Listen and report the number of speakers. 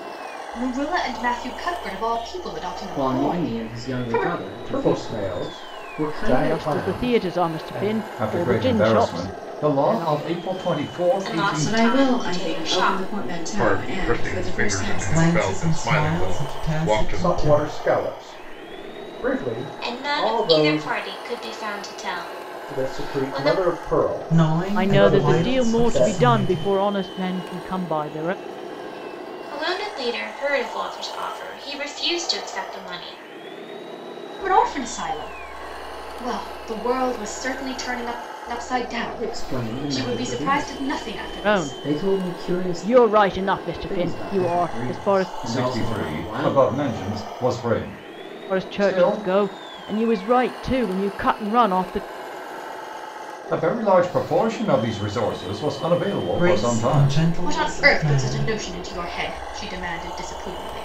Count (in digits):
9